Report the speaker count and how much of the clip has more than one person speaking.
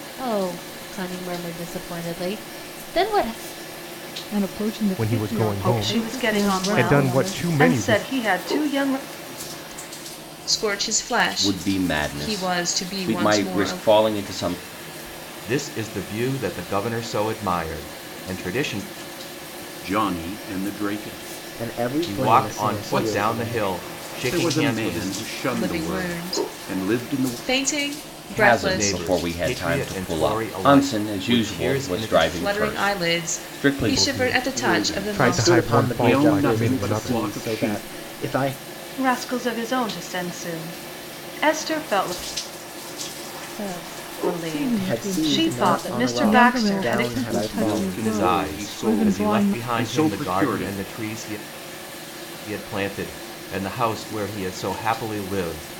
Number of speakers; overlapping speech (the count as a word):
nine, about 48%